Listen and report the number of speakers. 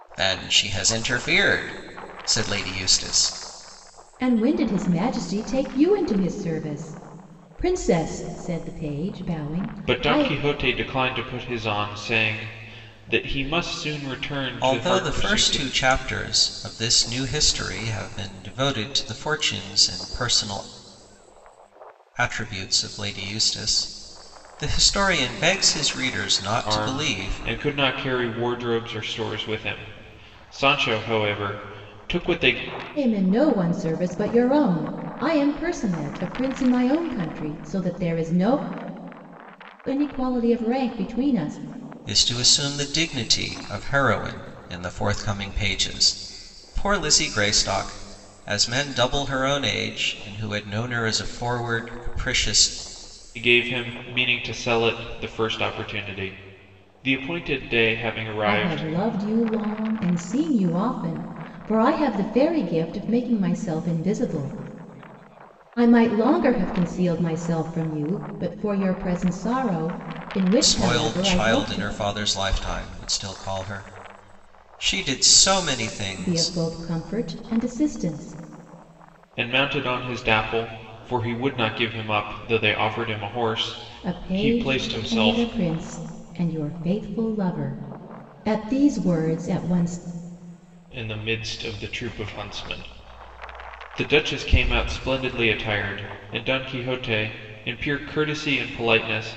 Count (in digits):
3